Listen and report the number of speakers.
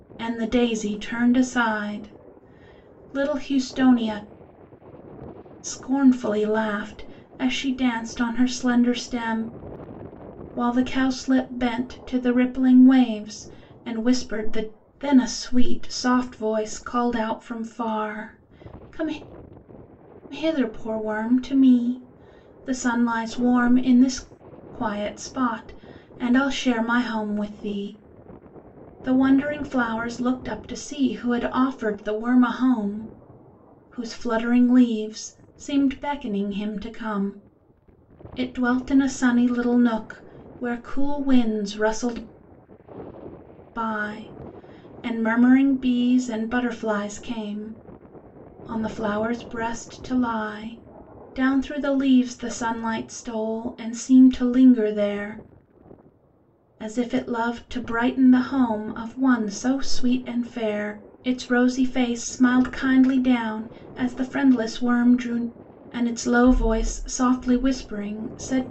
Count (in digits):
1